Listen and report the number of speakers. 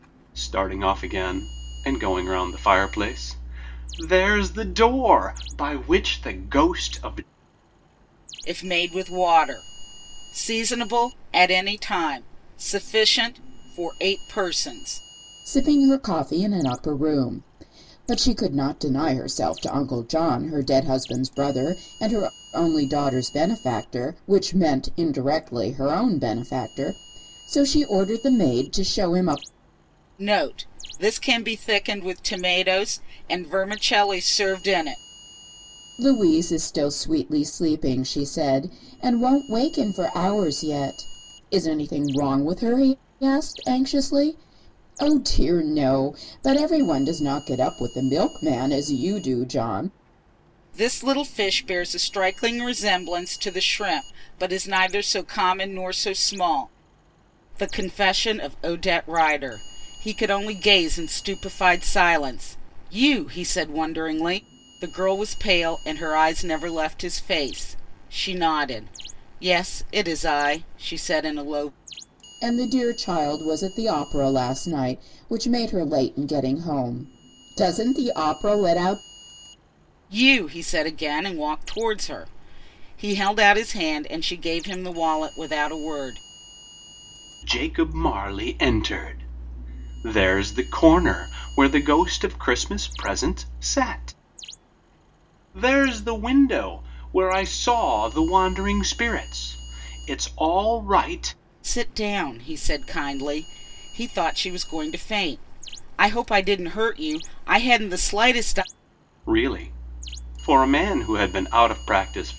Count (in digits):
3